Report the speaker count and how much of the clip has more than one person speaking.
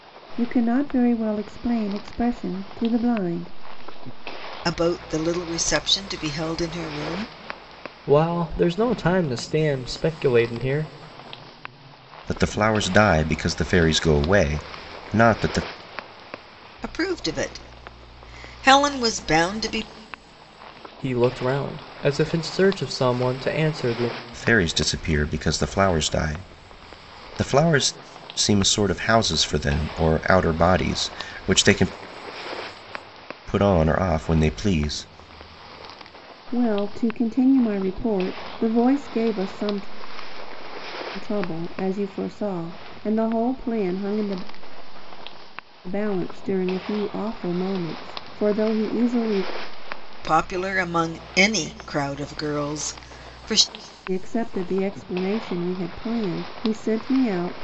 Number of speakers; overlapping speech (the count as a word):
four, no overlap